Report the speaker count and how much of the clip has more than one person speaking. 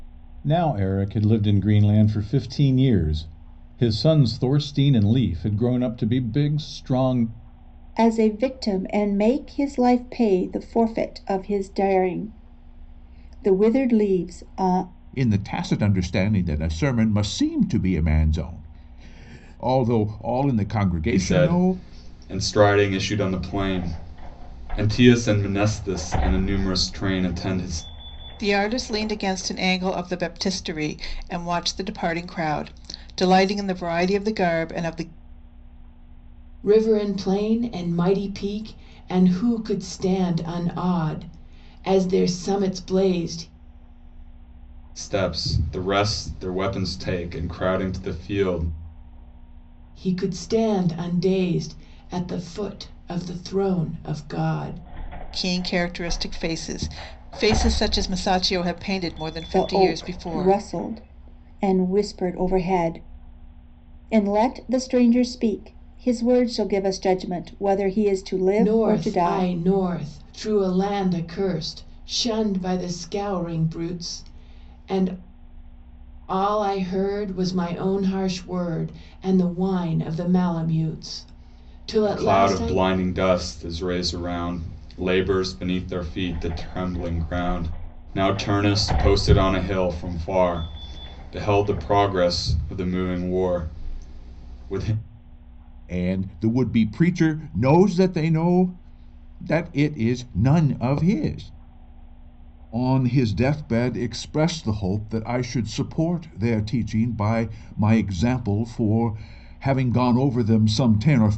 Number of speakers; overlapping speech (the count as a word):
six, about 3%